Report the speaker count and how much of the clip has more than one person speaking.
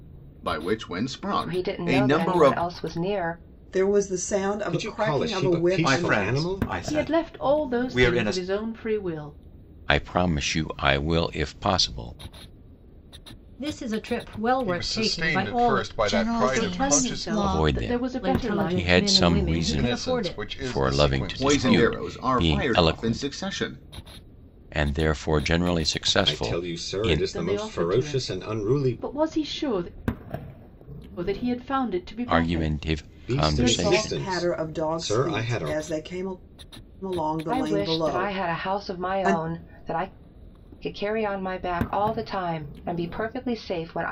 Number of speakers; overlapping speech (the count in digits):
10, about 49%